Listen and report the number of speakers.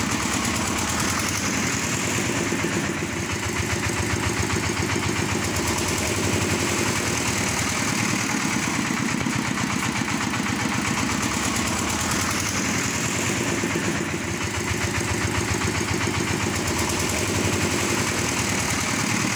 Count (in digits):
0